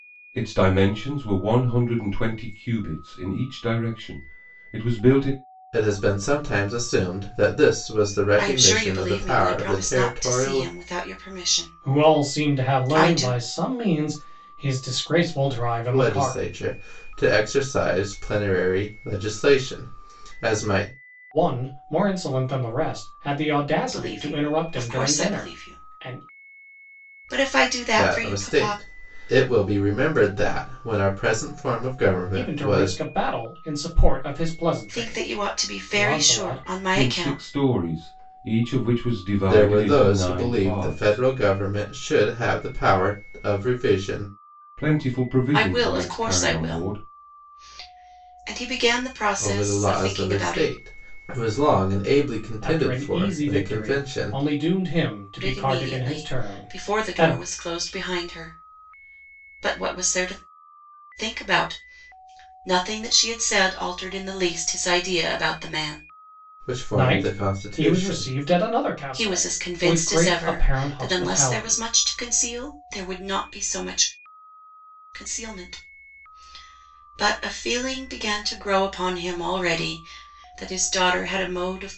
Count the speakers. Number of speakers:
four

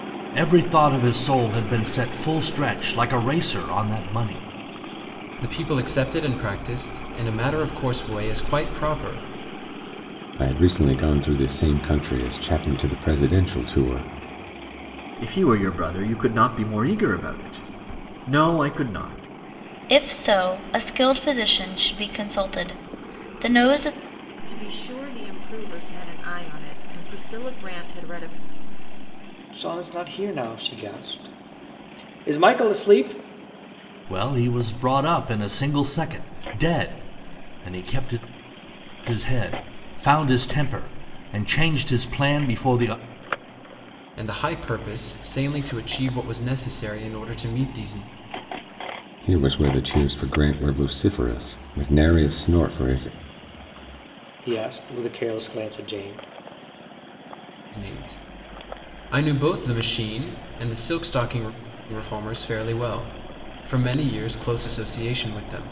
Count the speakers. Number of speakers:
seven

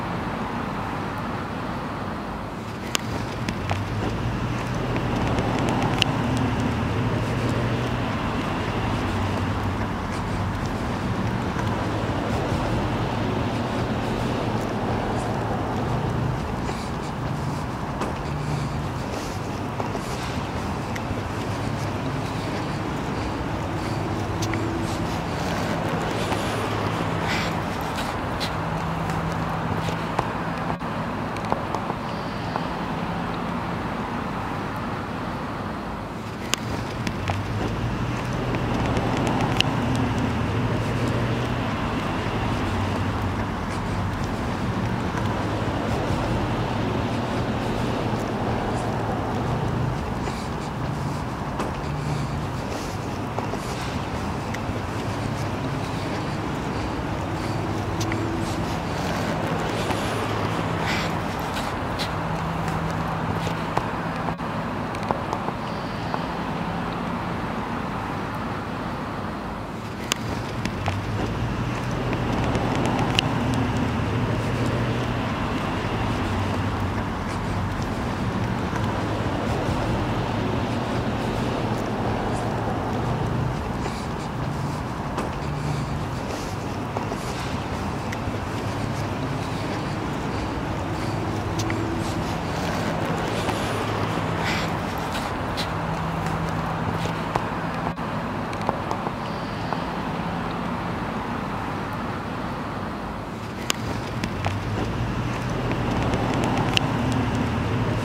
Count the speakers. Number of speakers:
zero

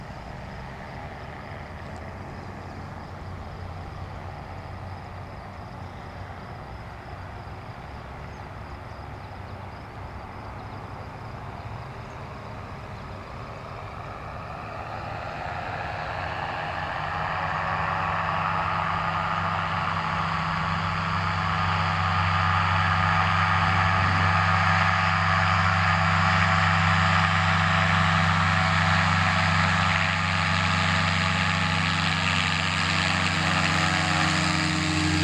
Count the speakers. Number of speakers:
zero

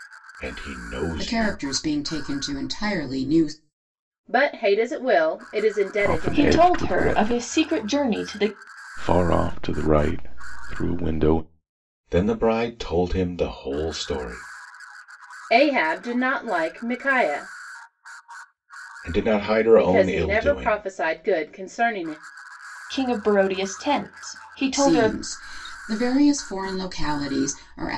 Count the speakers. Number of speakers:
five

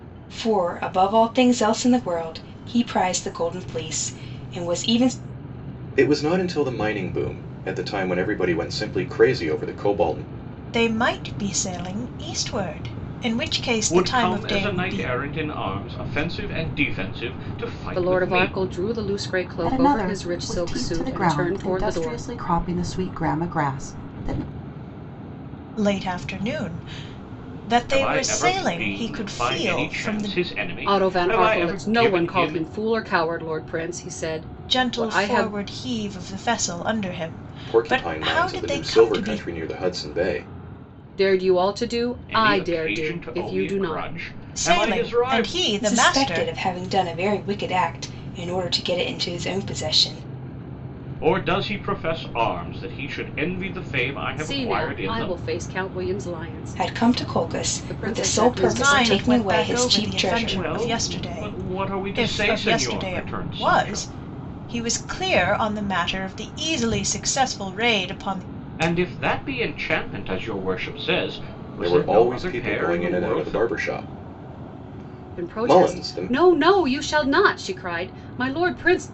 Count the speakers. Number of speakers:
six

